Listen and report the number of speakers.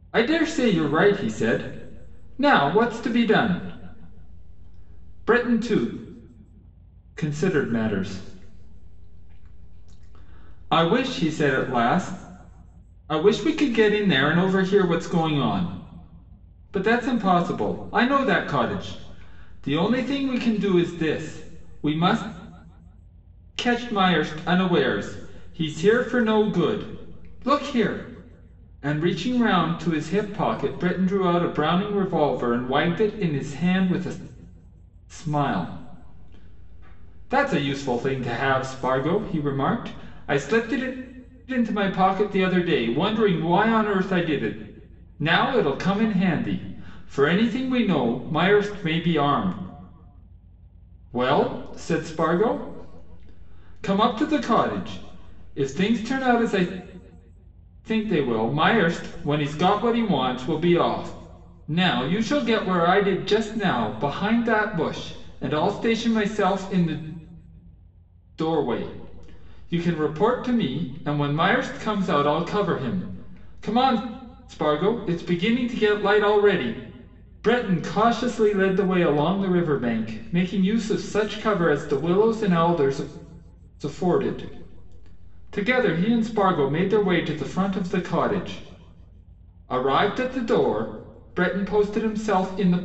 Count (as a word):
one